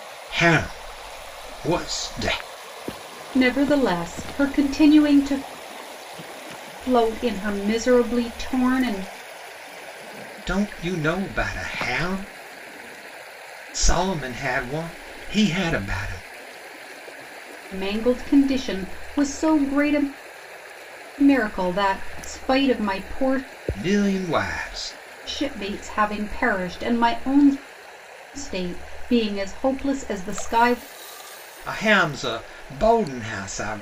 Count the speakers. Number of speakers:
two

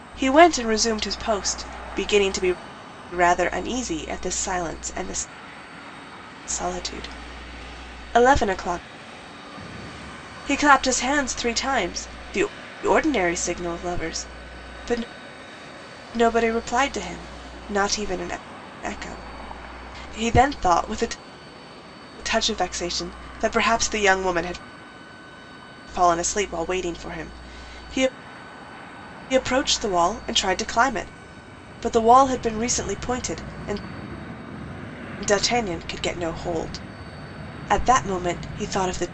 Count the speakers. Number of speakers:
one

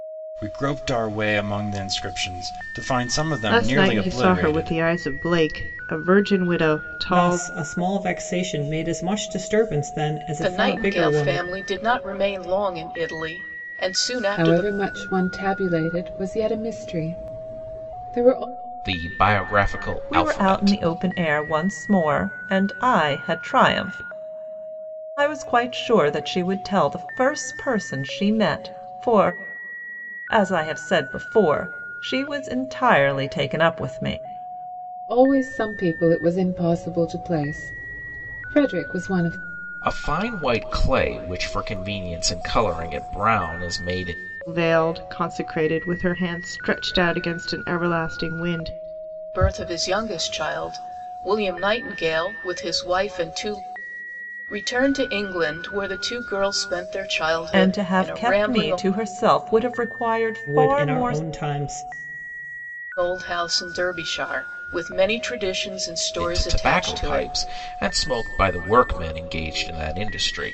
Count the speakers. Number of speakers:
seven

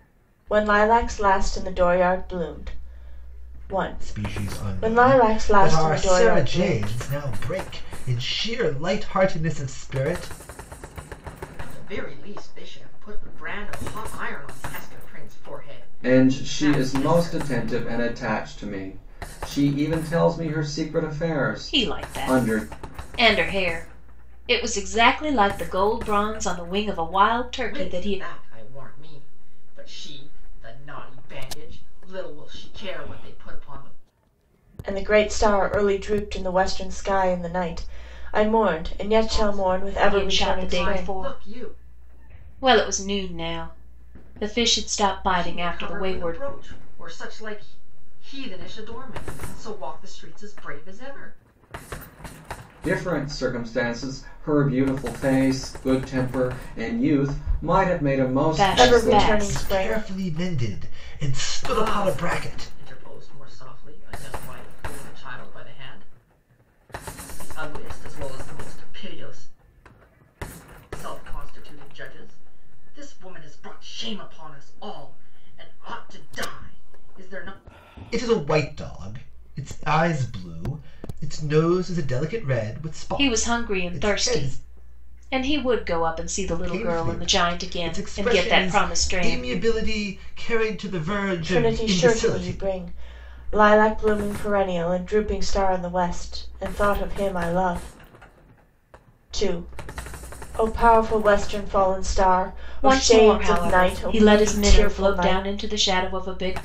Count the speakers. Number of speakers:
five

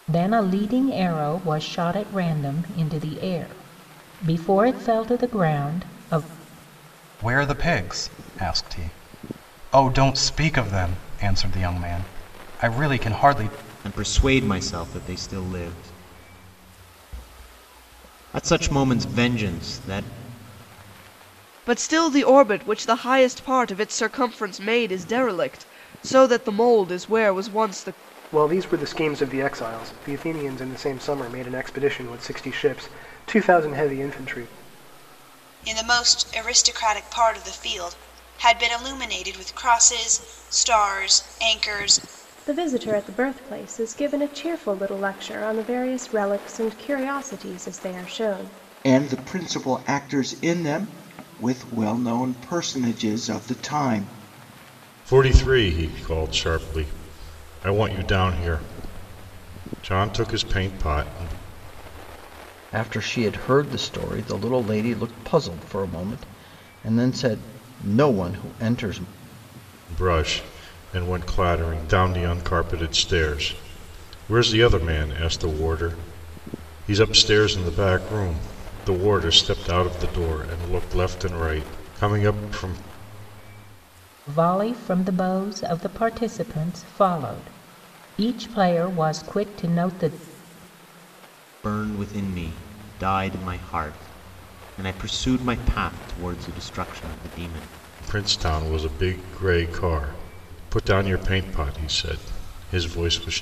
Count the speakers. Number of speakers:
ten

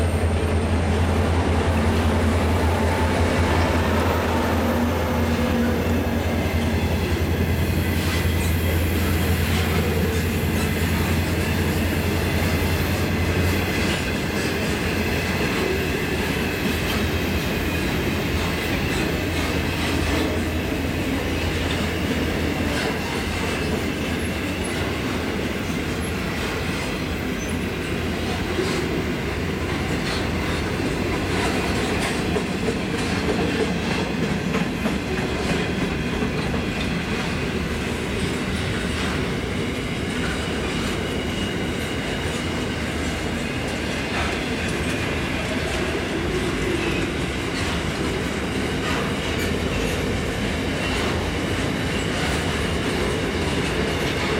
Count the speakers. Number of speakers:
zero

